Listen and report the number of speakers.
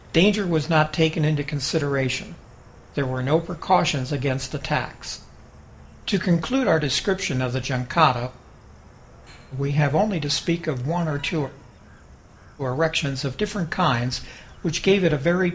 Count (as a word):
one